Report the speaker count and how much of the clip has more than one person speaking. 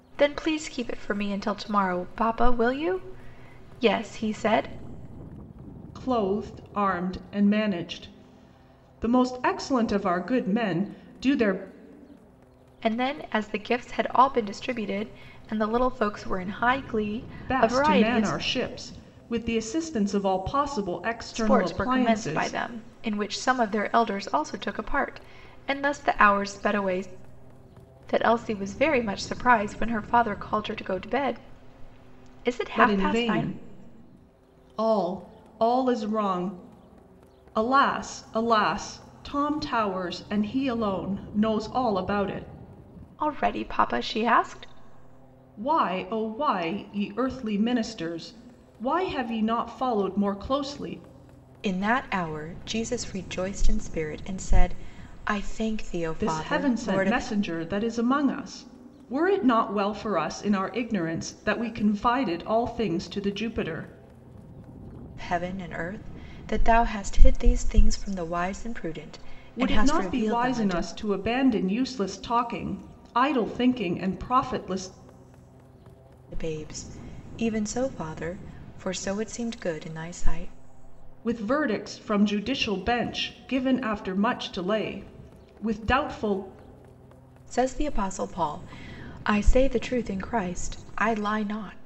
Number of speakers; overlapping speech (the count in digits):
2, about 6%